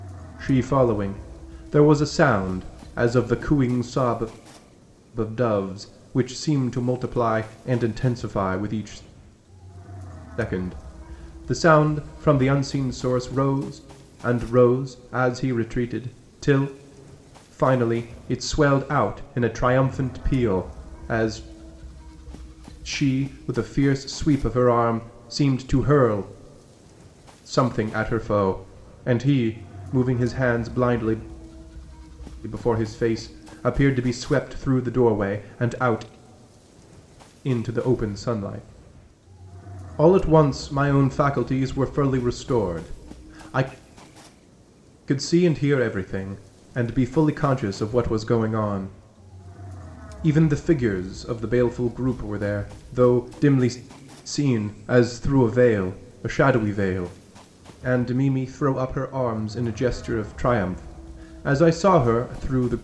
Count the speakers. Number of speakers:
1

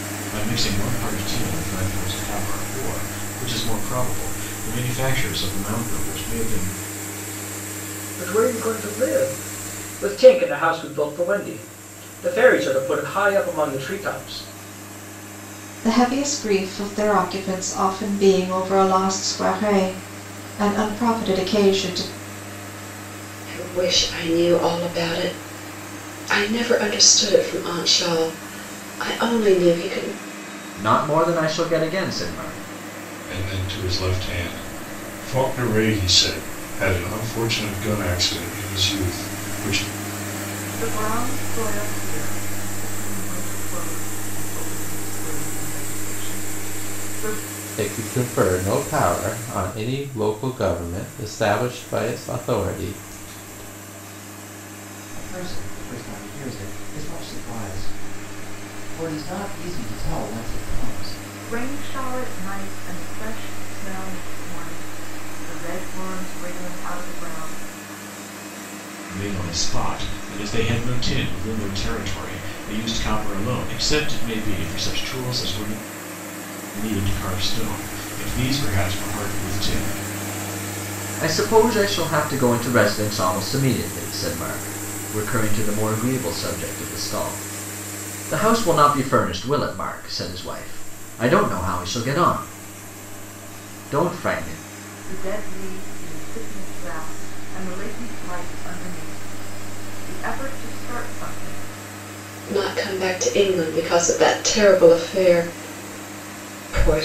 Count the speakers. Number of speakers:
9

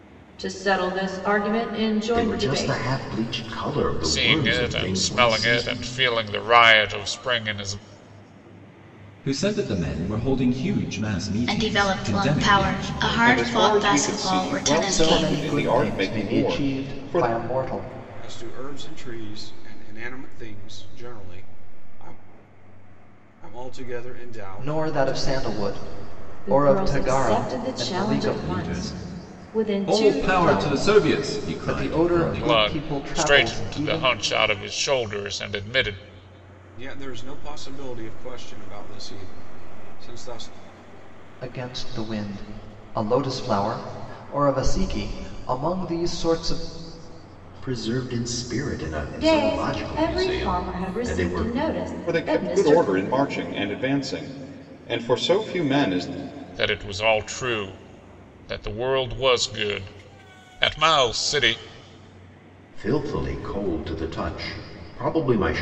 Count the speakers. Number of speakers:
8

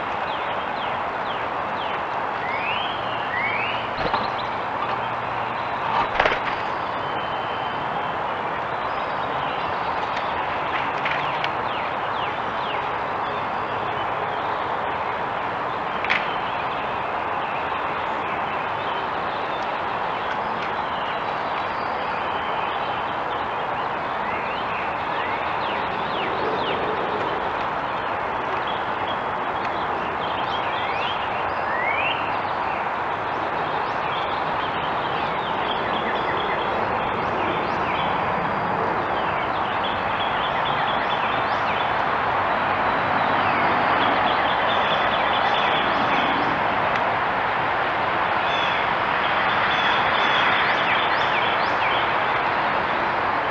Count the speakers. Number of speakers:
0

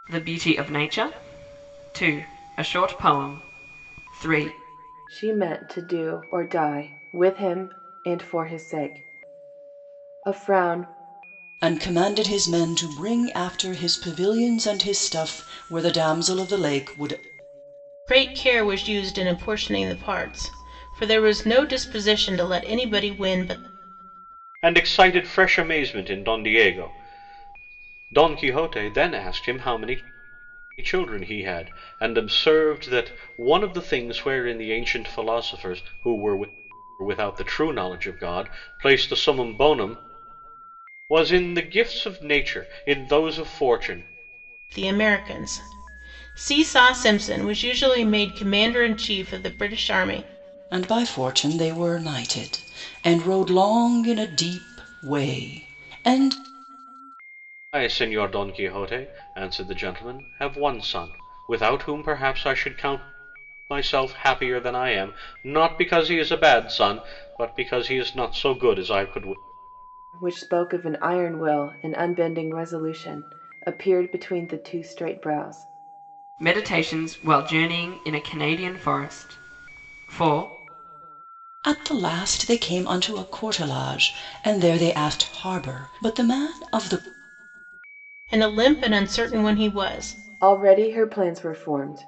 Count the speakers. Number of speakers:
5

